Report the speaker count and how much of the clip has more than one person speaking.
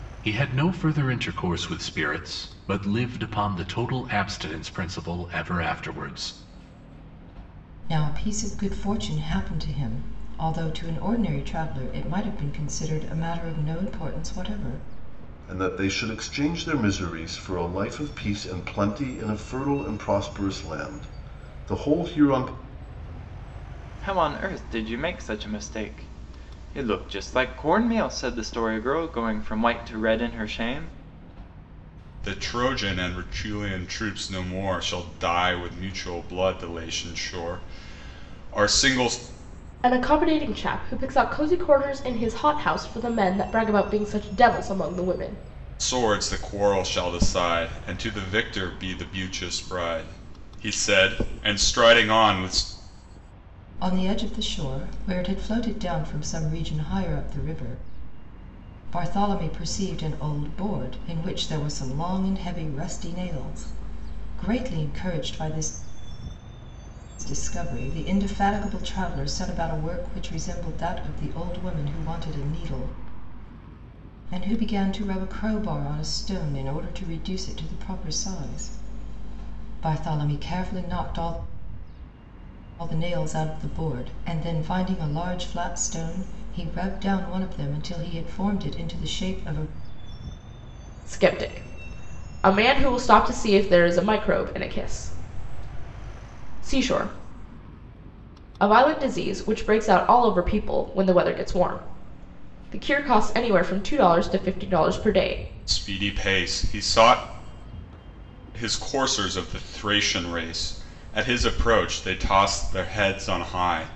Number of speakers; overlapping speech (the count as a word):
six, no overlap